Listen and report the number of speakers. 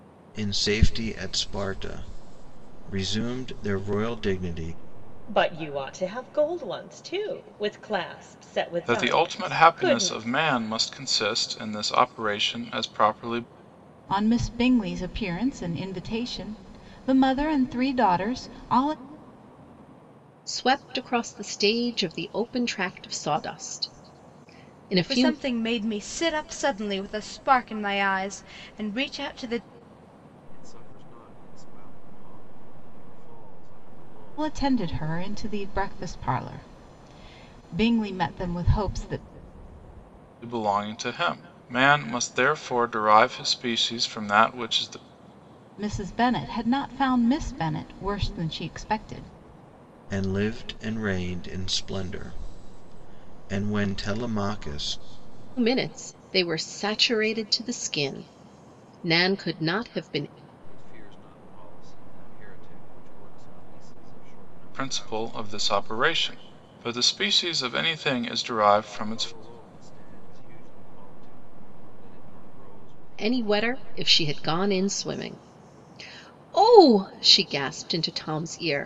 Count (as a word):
seven